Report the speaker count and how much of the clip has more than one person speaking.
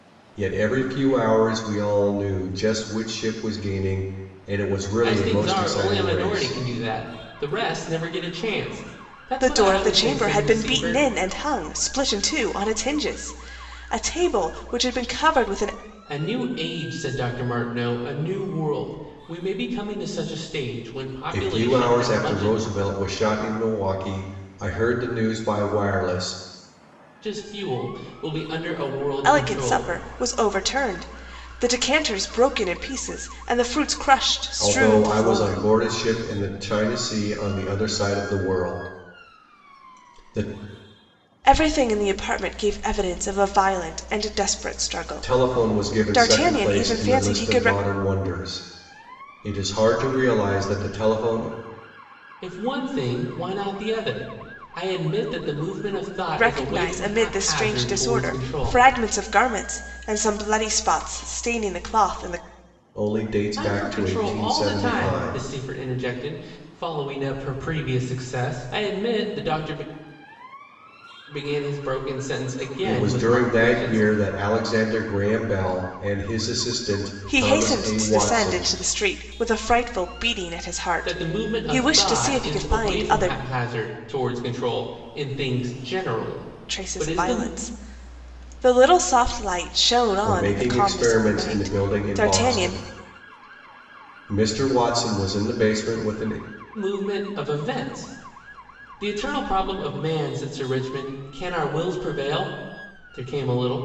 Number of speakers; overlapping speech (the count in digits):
3, about 21%